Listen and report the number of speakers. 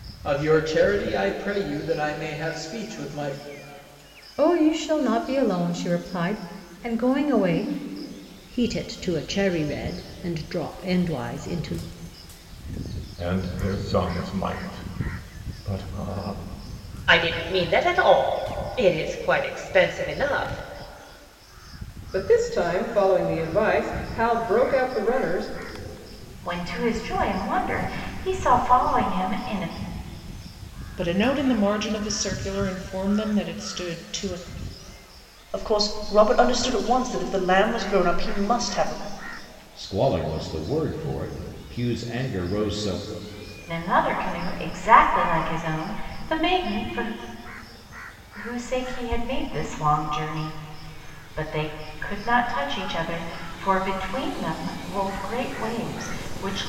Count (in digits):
10